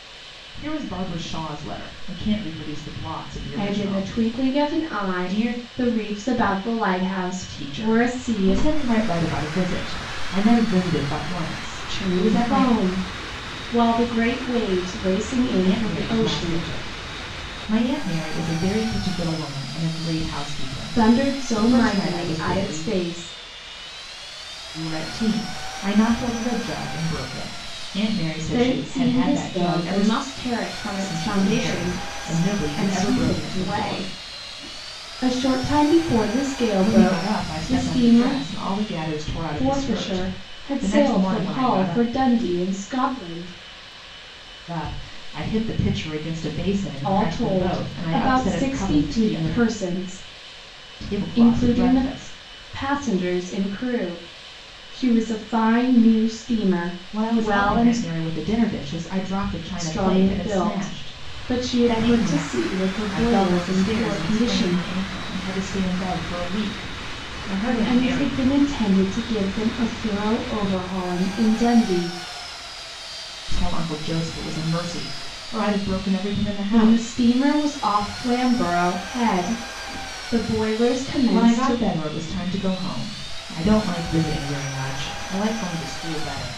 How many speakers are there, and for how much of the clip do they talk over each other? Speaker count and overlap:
two, about 31%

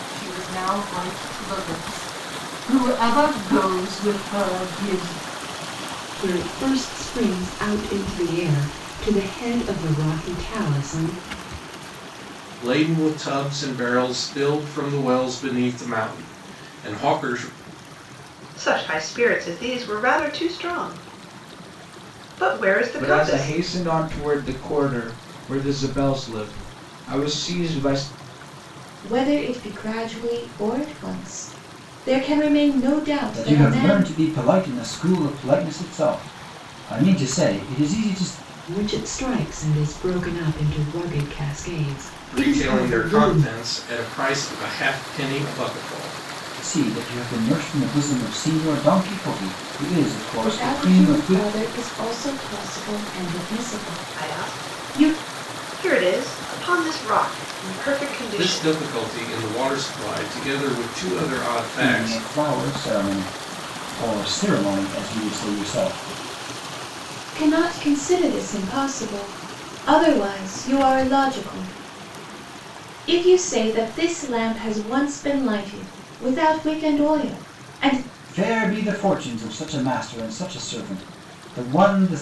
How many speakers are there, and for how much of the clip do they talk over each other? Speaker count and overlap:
seven, about 7%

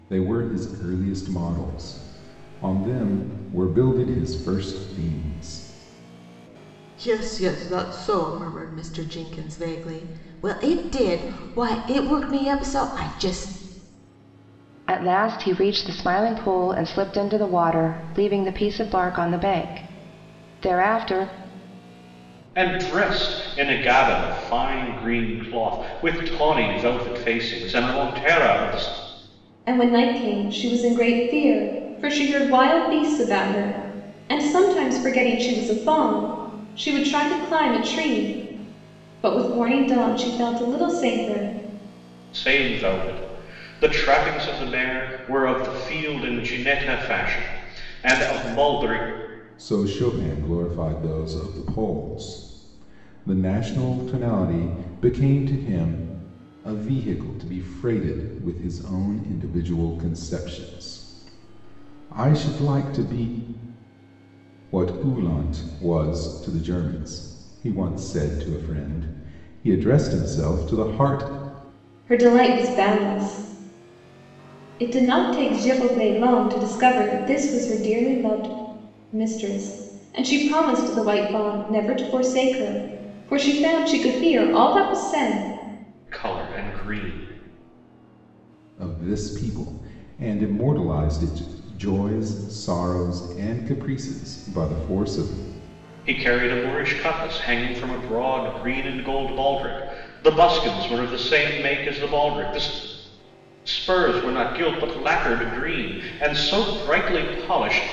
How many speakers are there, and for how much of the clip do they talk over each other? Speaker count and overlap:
five, no overlap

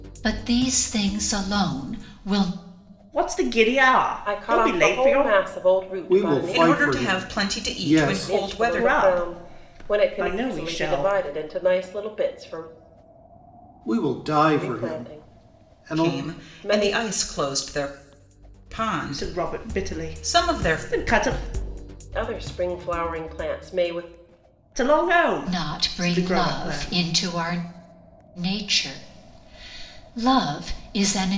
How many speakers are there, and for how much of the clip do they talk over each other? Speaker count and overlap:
five, about 38%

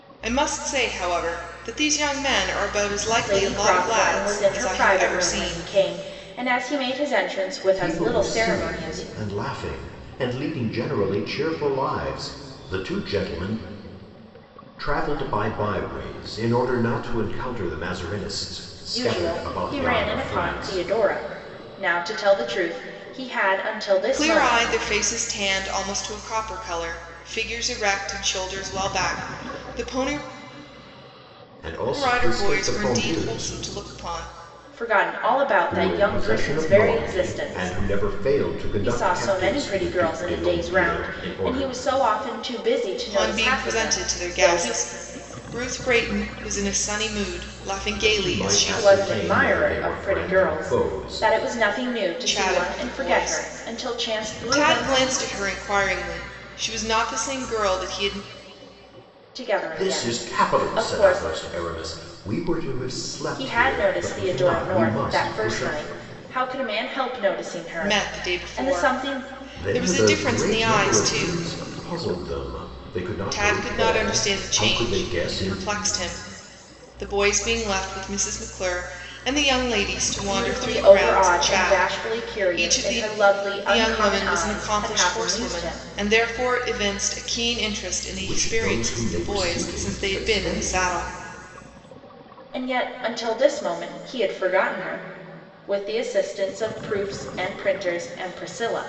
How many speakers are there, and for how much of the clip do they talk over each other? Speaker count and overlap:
three, about 39%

